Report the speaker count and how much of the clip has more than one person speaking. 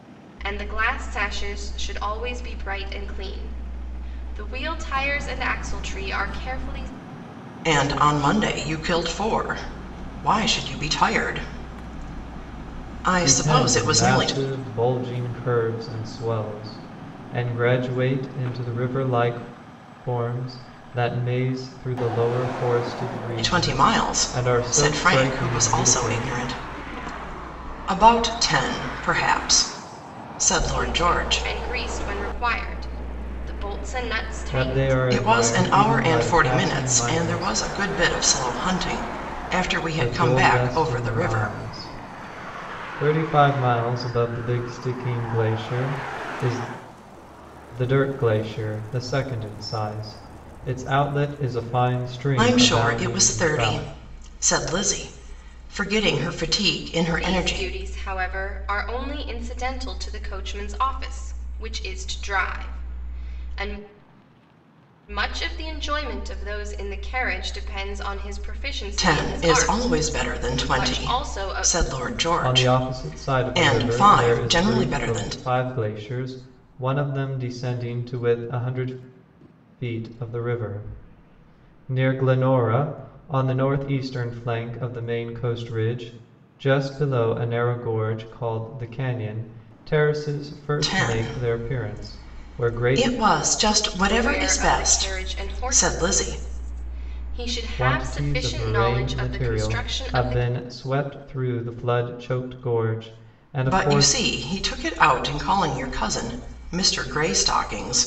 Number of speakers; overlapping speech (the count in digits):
3, about 24%